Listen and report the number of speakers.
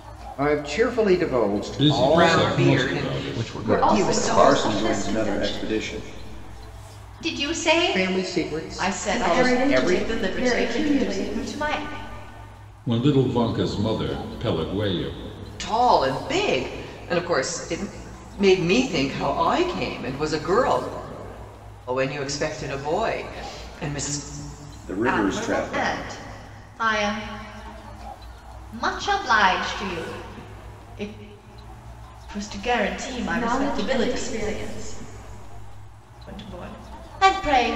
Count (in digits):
7